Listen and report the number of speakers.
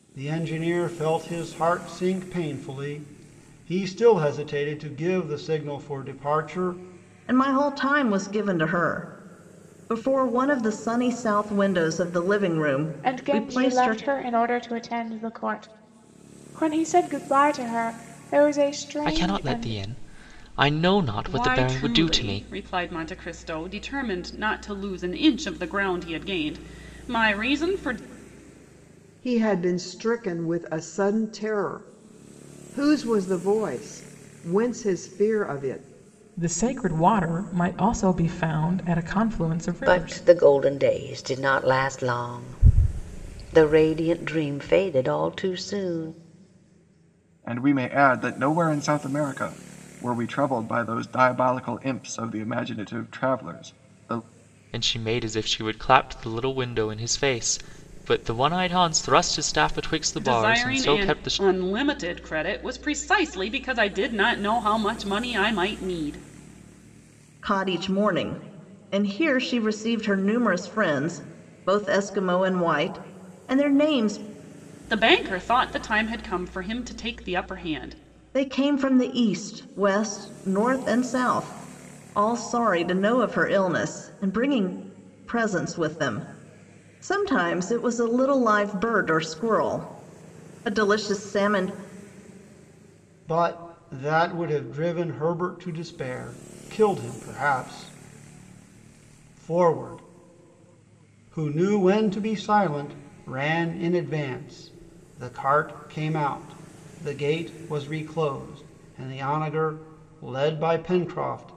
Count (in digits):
9